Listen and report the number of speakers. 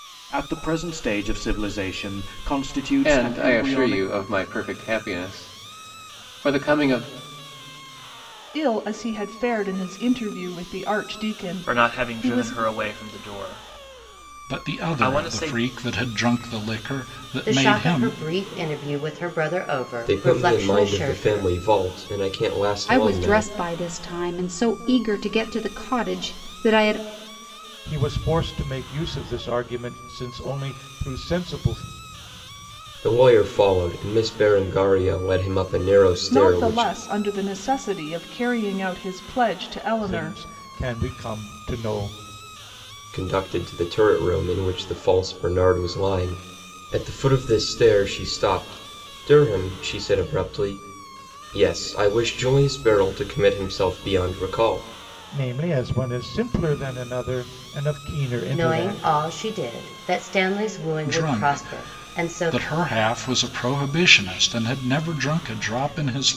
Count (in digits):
9